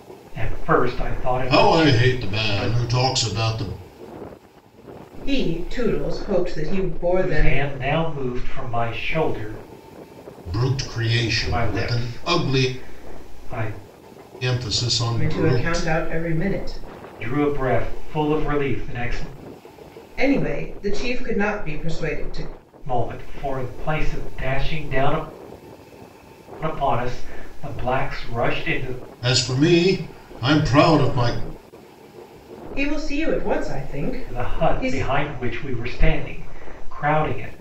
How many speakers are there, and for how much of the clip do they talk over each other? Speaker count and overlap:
3, about 14%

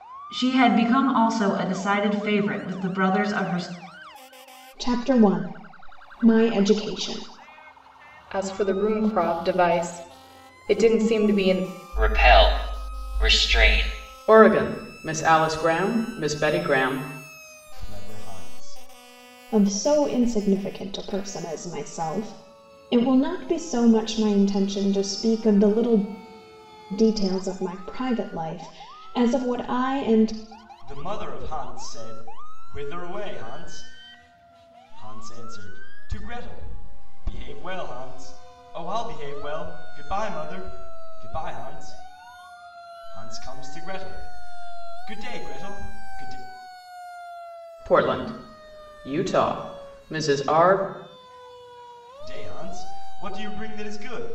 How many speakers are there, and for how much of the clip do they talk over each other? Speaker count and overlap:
6, no overlap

